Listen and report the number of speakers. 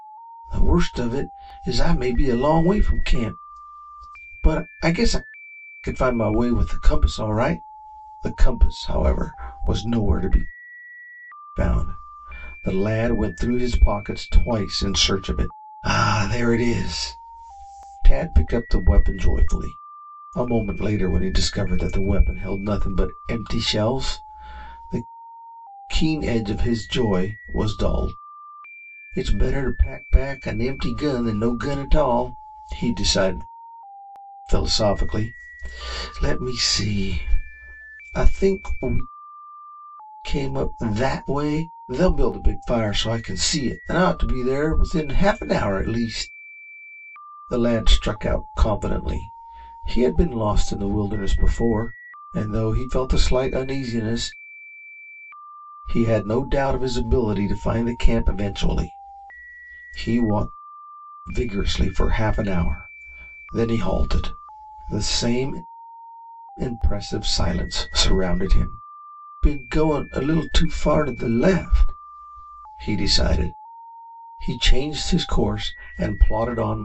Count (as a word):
one